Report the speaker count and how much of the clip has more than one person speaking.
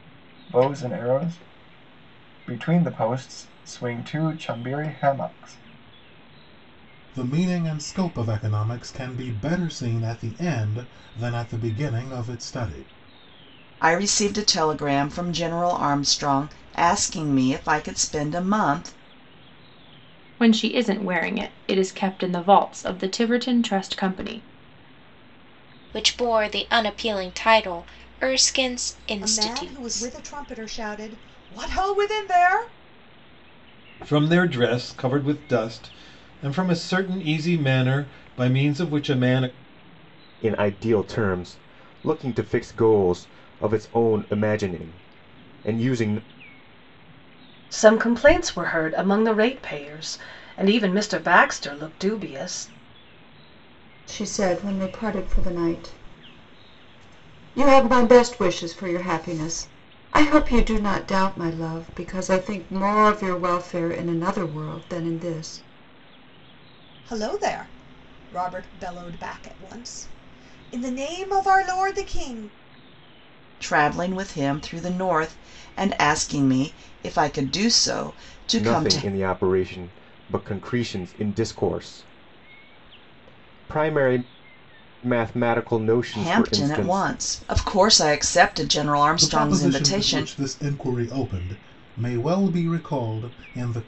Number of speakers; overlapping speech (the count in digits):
10, about 4%